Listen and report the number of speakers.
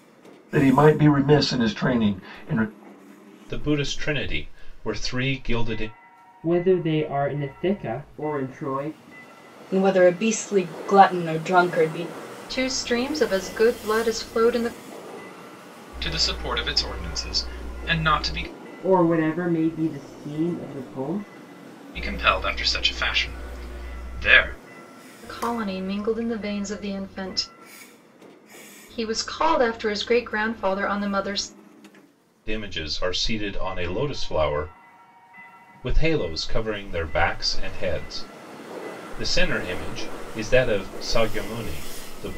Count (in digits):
6